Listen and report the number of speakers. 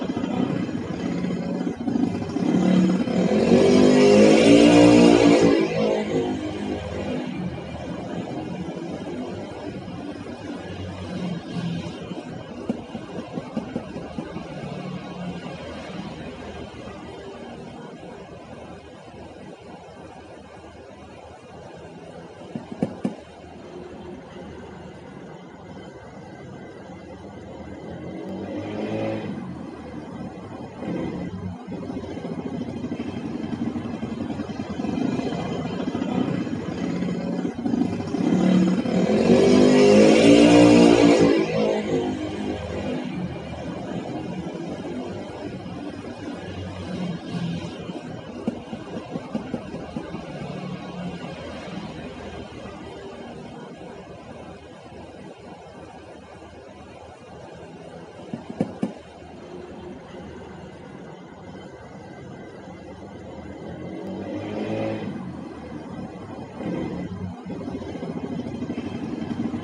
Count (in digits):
0